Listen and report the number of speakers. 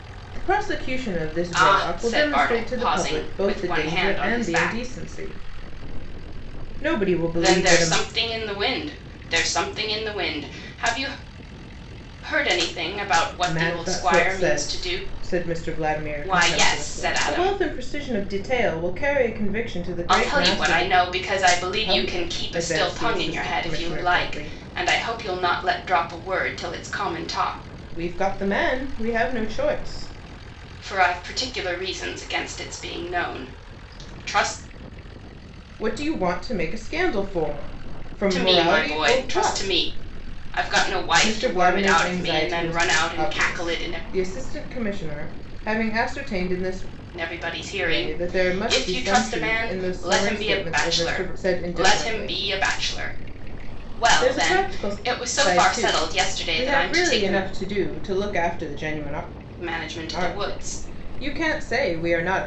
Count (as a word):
two